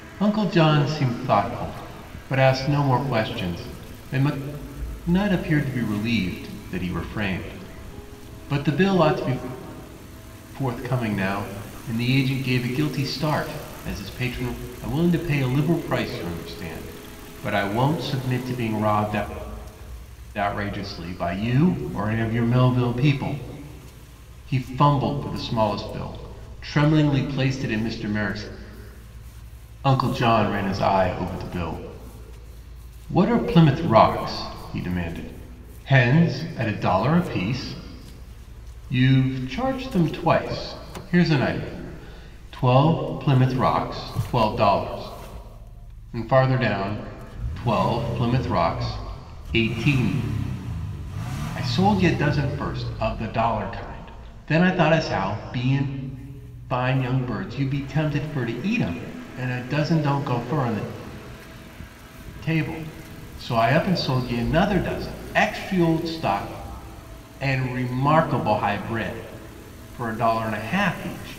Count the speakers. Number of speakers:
1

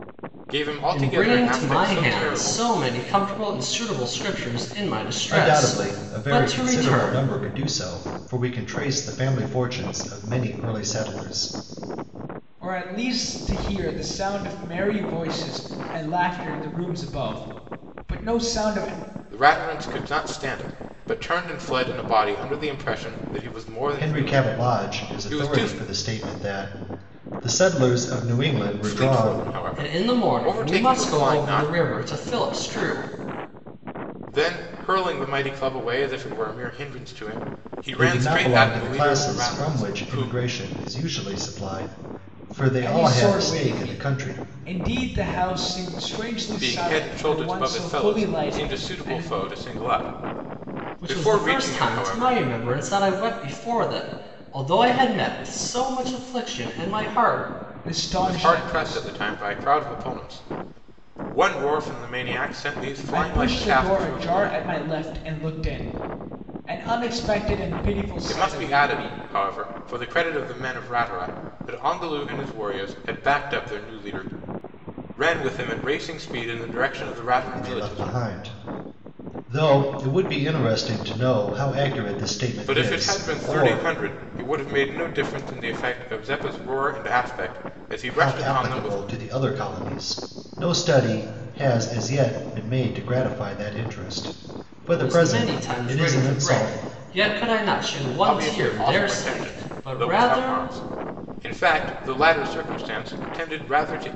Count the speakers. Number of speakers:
4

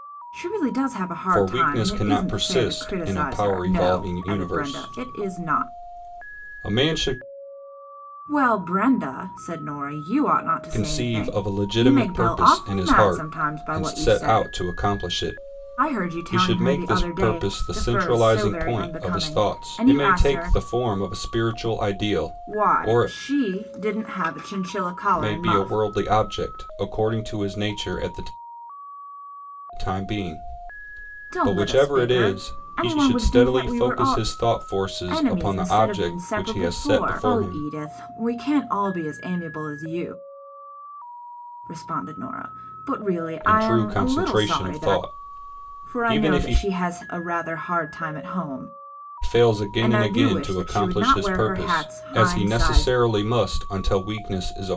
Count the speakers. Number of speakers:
2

